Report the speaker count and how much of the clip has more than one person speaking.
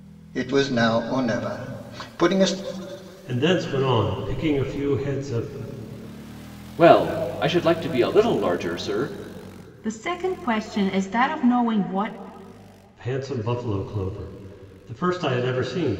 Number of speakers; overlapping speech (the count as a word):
four, no overlap